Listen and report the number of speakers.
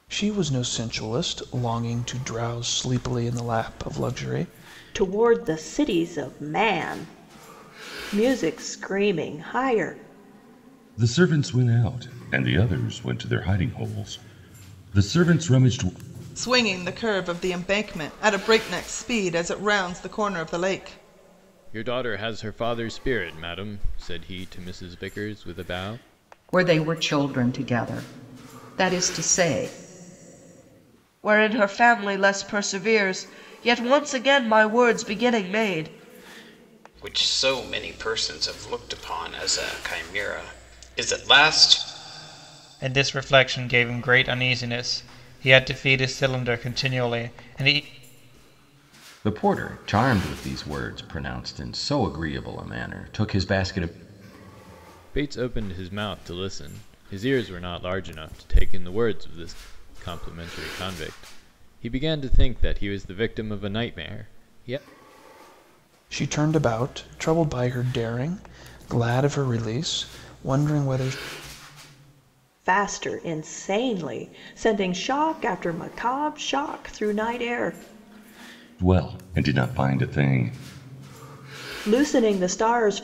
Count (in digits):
10